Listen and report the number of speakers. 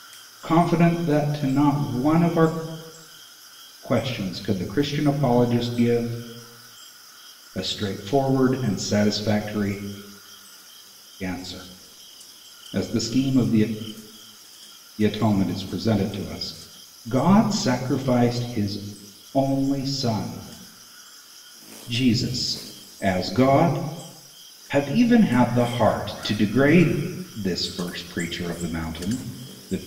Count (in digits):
1